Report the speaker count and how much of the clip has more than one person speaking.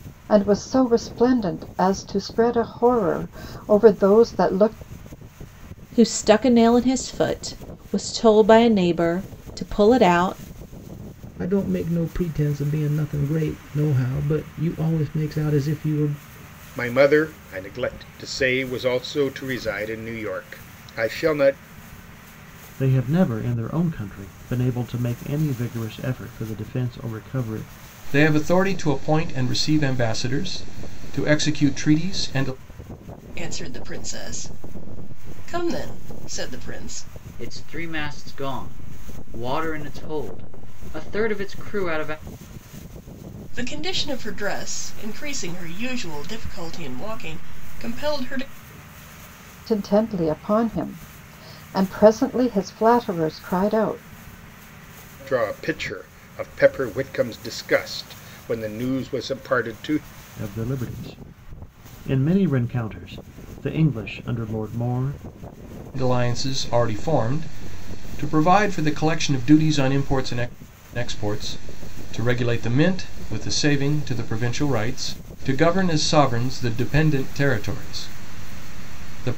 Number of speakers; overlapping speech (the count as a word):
eight, no overlap